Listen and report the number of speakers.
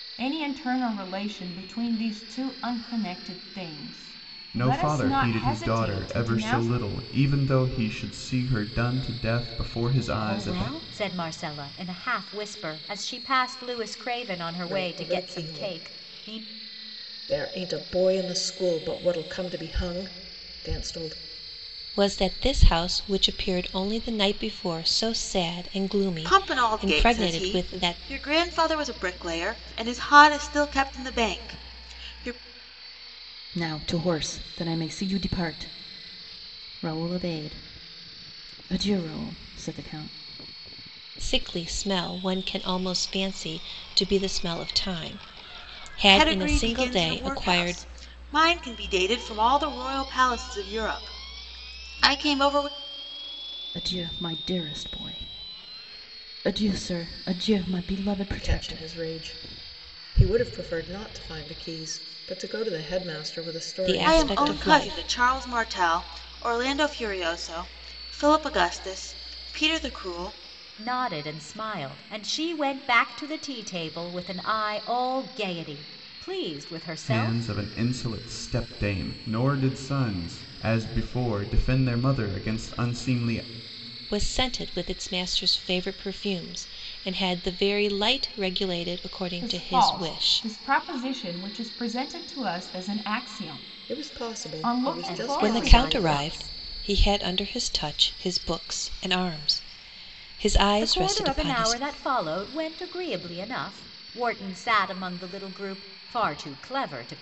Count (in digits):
7